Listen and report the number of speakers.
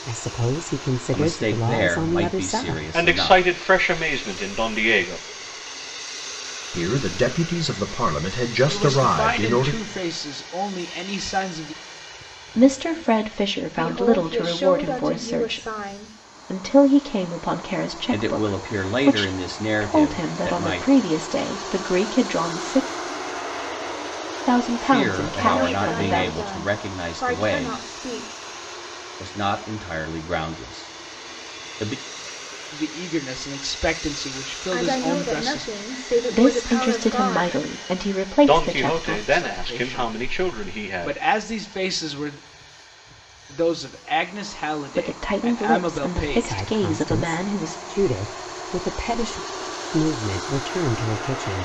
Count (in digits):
7